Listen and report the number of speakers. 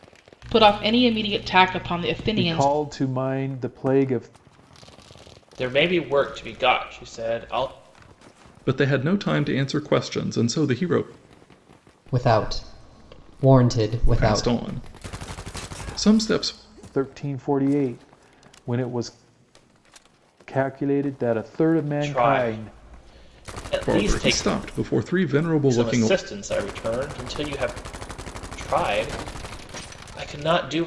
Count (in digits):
5